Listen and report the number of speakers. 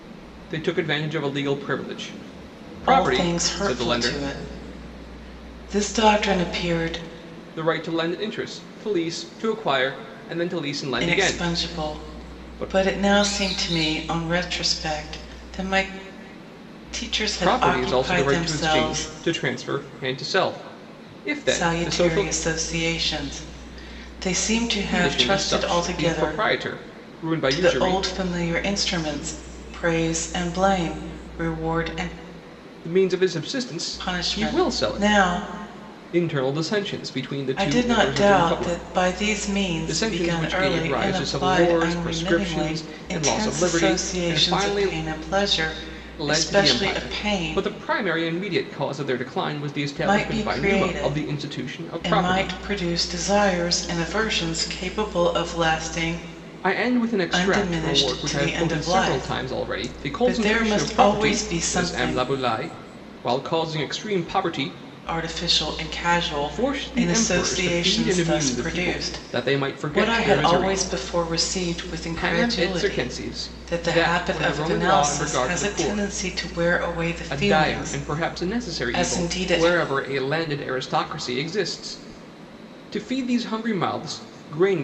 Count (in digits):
2